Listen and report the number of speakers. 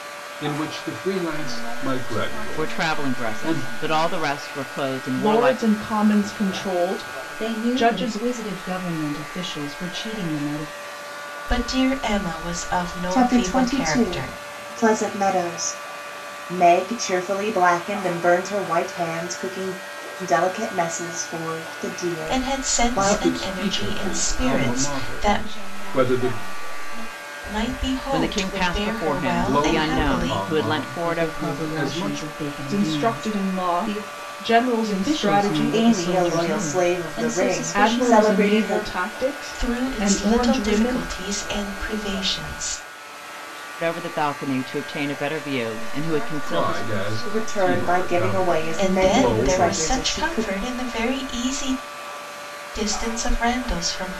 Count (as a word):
seven